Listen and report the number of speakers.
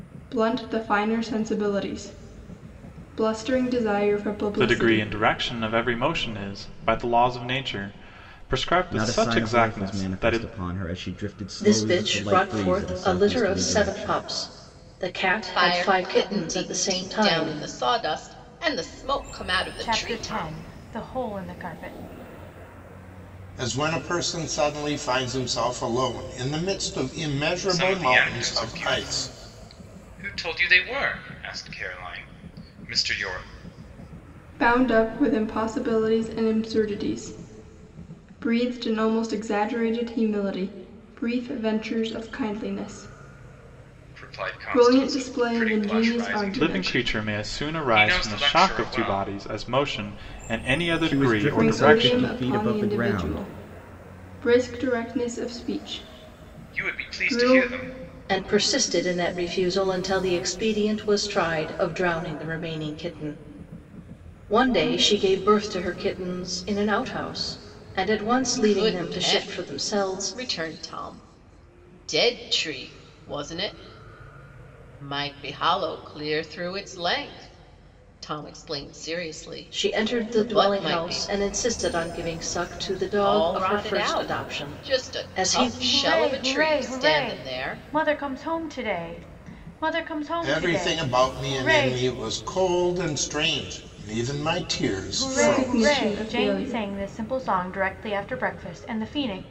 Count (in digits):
8